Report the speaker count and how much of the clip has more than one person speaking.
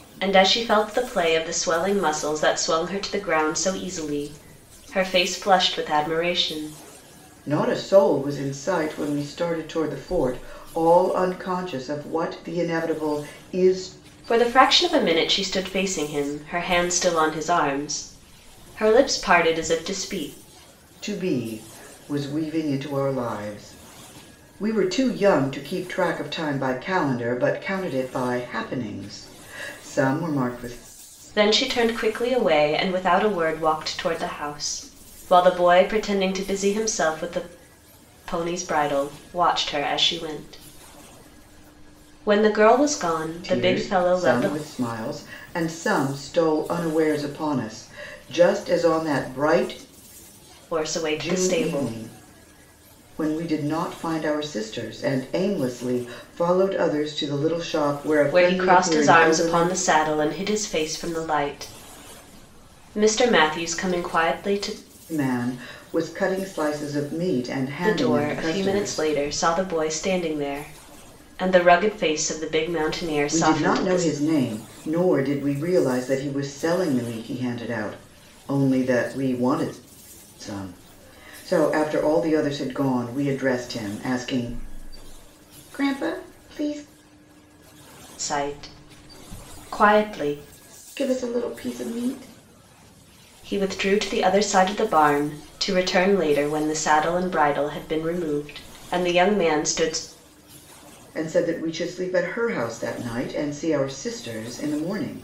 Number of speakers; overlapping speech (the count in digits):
2, about 5%